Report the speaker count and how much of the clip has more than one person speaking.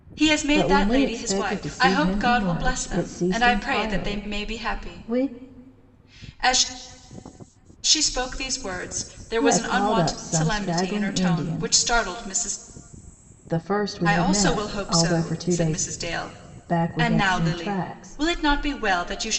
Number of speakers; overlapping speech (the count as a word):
two, about 53%